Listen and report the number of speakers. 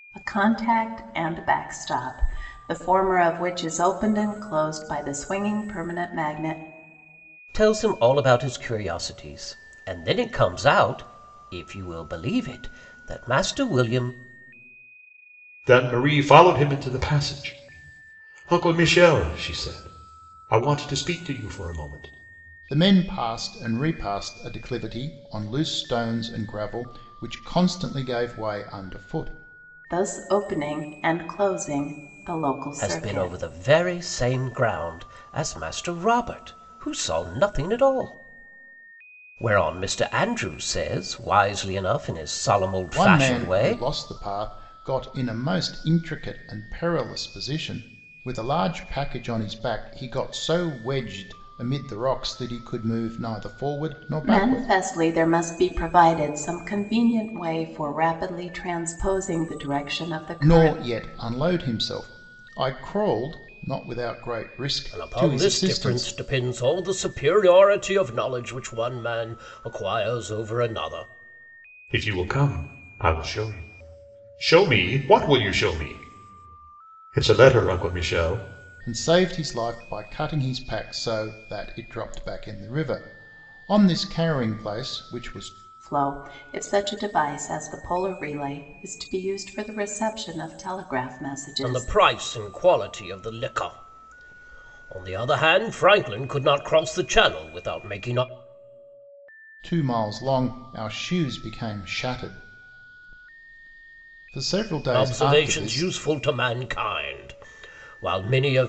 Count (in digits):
4